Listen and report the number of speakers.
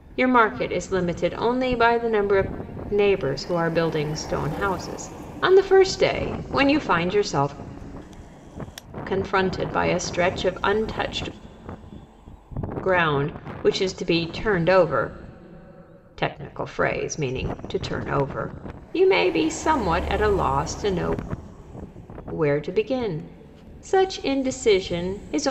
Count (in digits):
1